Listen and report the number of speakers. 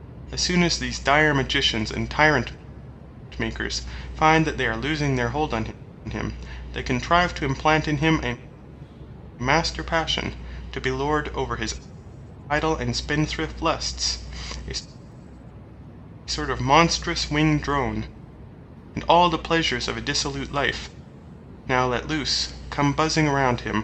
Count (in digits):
1